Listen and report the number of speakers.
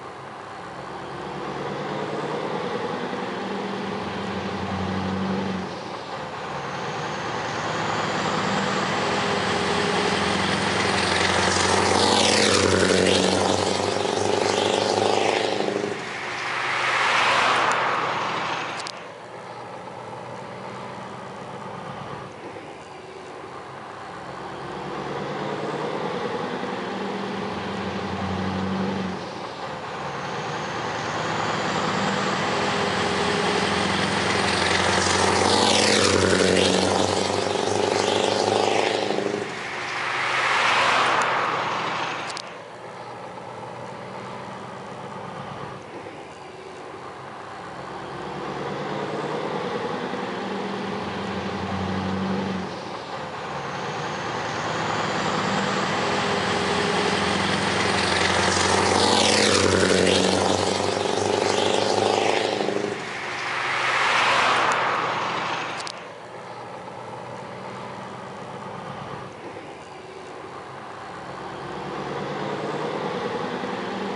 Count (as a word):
zero